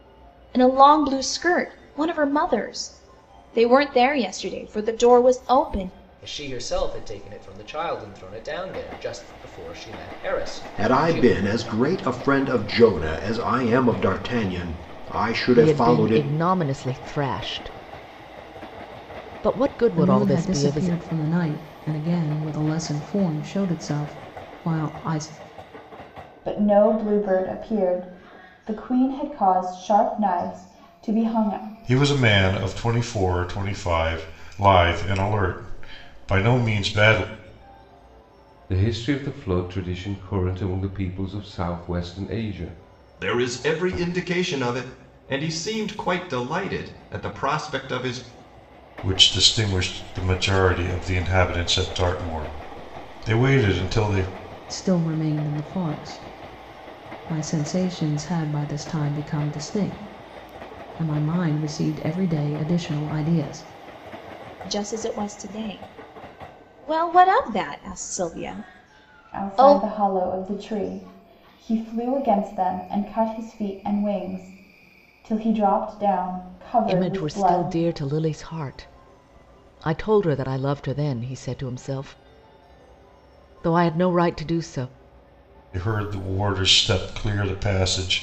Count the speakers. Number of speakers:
nine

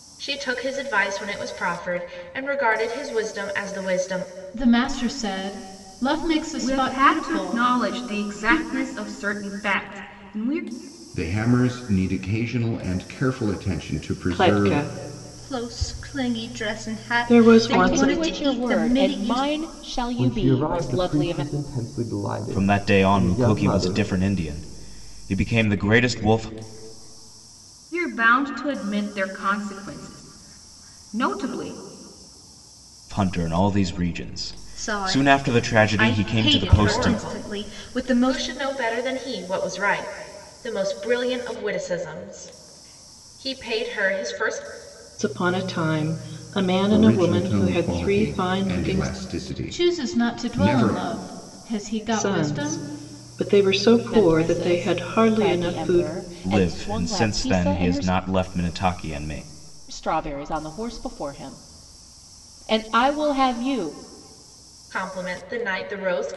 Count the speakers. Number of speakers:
nine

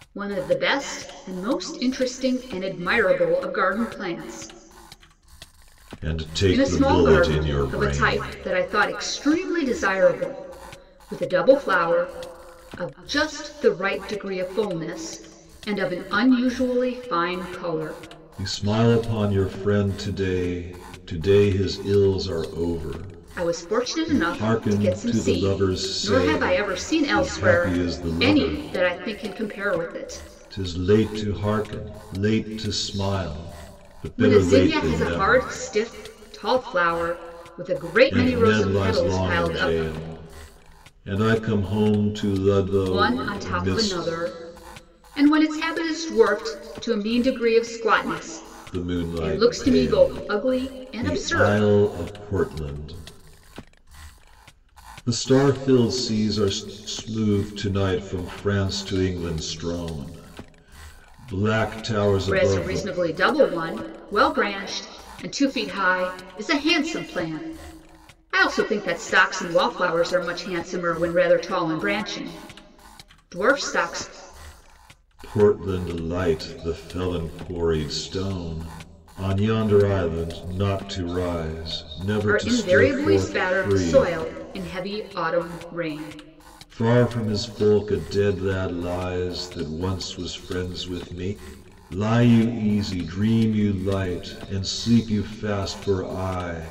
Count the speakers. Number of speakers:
two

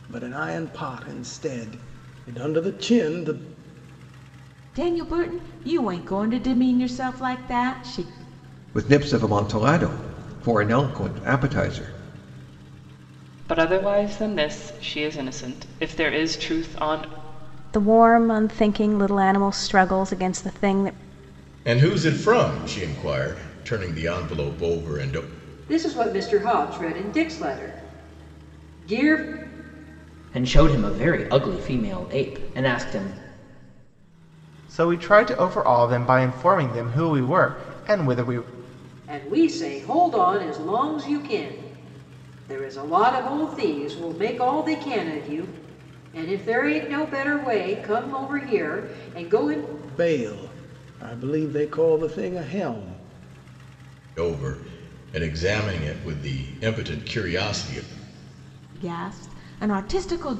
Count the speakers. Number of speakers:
nine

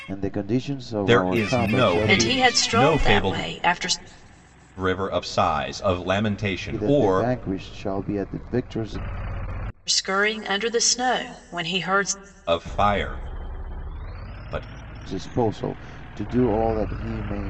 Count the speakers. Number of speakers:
three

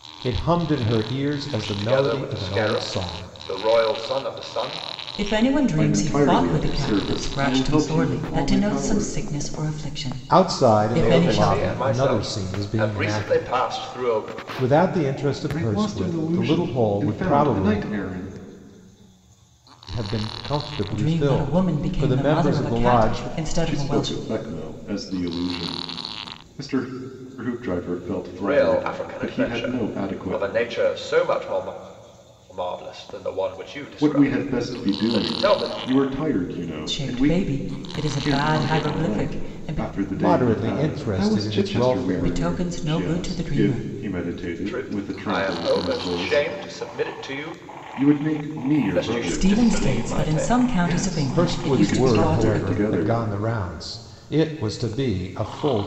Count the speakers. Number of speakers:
four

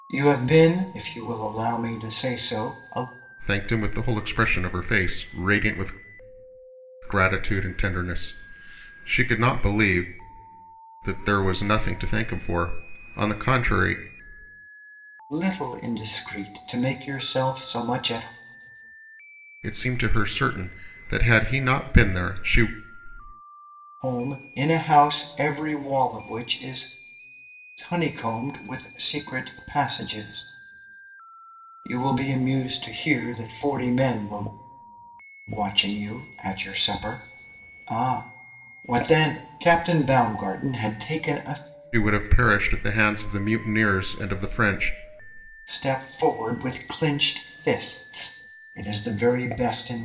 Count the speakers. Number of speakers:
two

